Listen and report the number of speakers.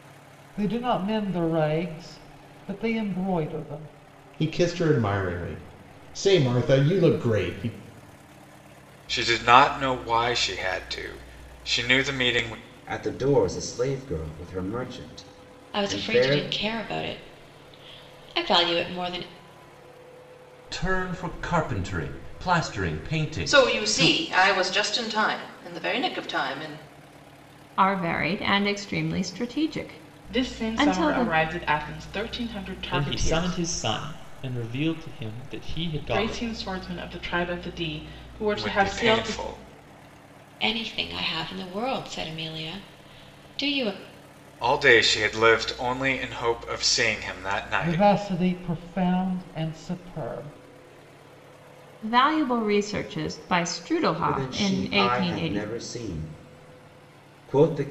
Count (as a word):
ten